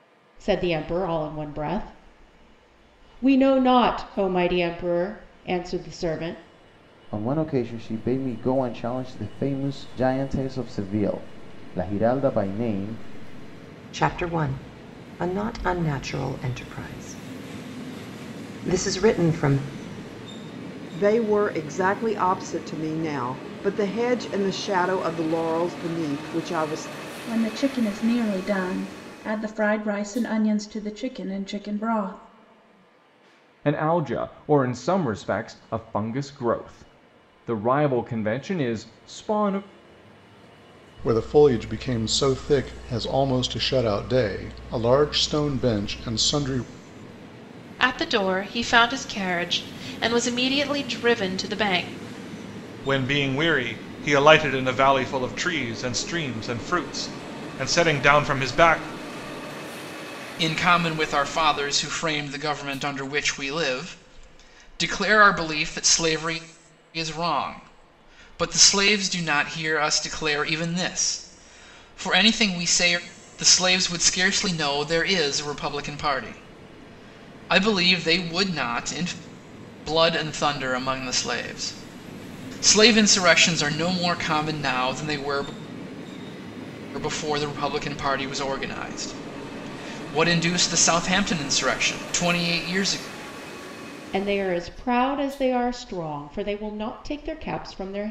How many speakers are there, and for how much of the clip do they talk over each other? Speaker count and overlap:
ten, no overlap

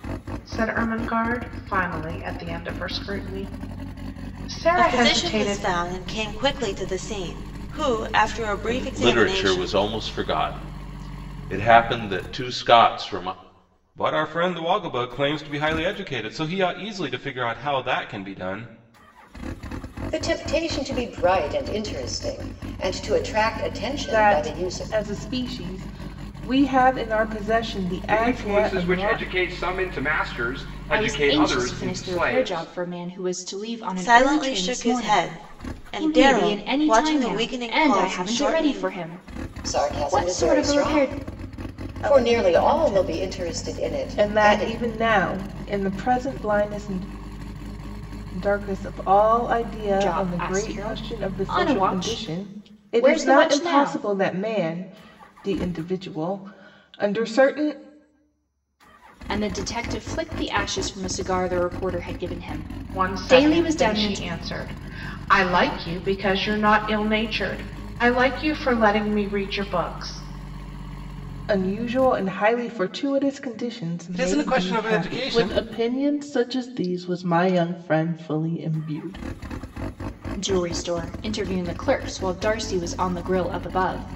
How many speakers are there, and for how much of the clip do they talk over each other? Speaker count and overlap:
eight, about 26%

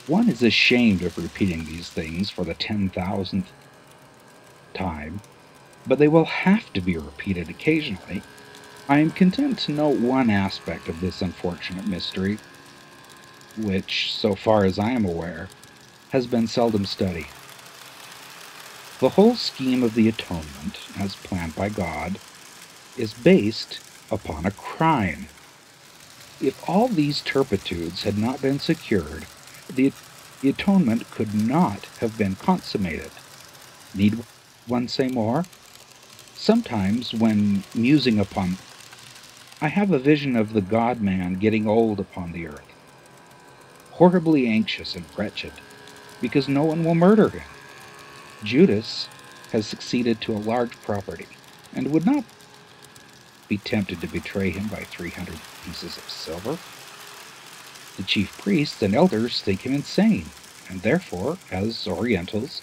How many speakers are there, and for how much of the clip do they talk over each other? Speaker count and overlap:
one, no overlap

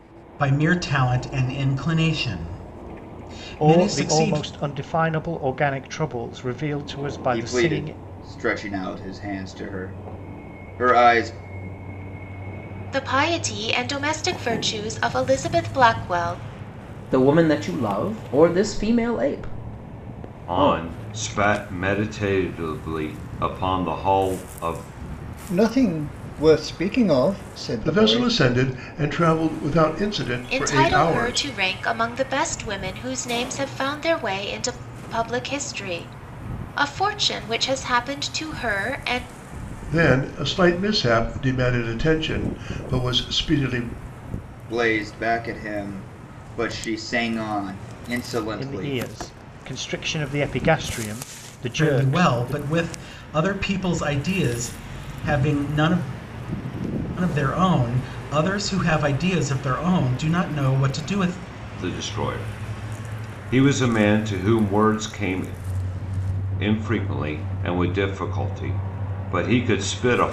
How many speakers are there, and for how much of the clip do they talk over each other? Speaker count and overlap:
eight, about 7%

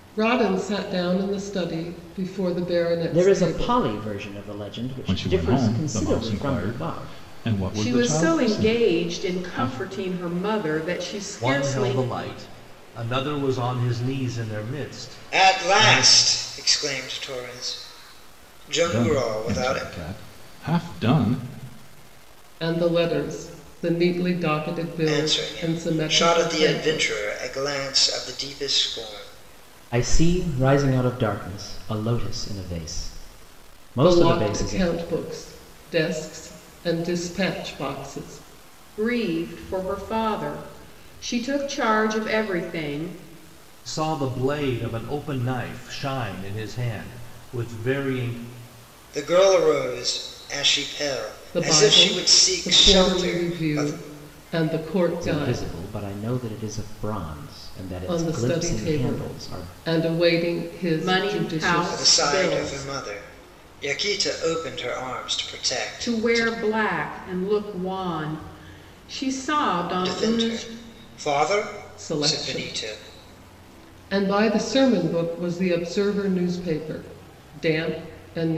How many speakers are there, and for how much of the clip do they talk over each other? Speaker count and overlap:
six, about 25%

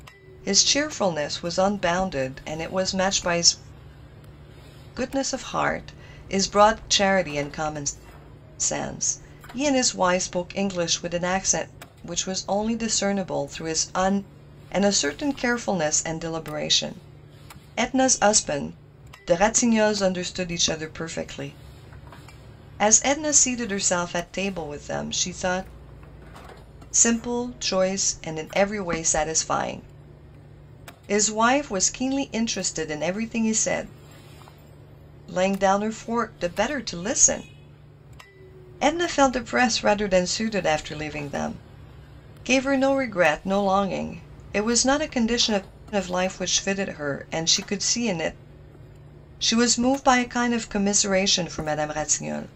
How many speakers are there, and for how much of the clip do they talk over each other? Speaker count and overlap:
one, no overlap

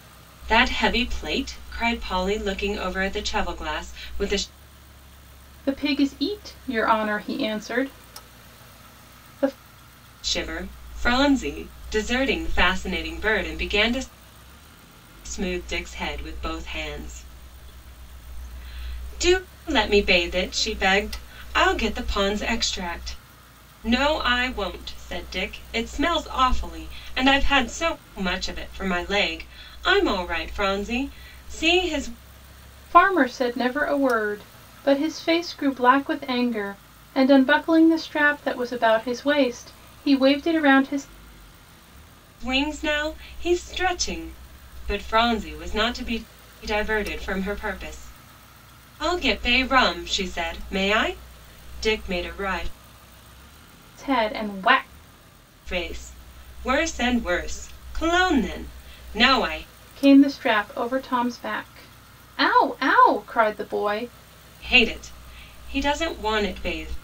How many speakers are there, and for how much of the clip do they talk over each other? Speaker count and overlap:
two, no overlap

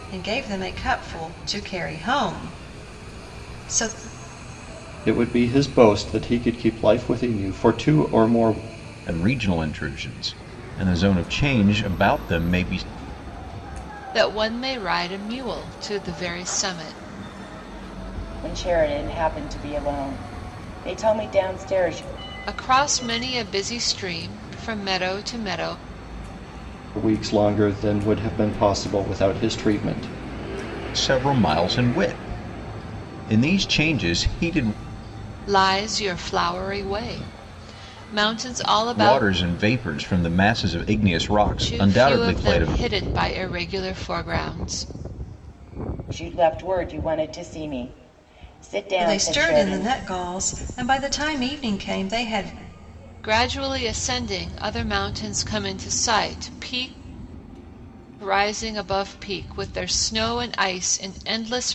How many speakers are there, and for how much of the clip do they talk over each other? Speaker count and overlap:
five, about 4%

